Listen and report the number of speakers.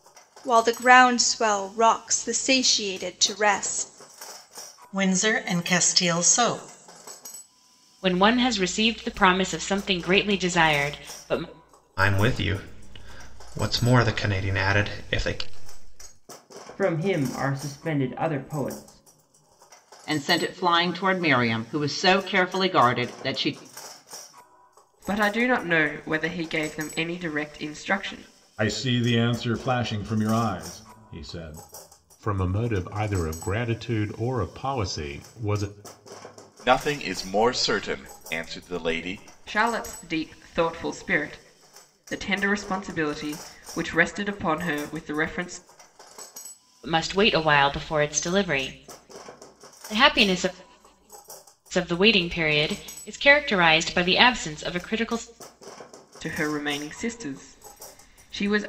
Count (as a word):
ten